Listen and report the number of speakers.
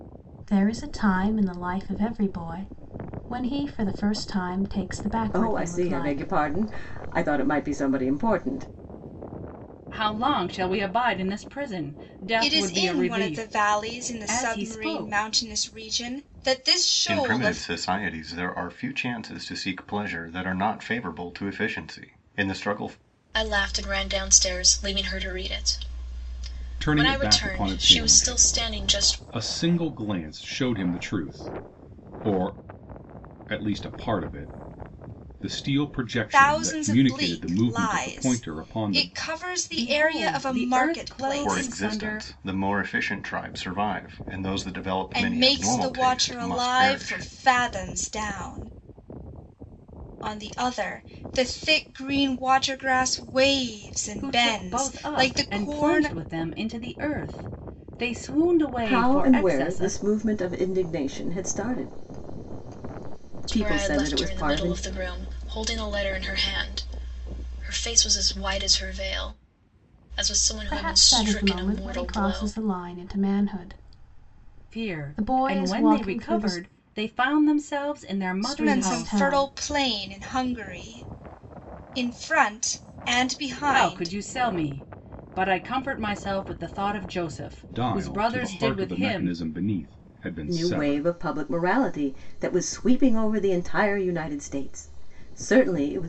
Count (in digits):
7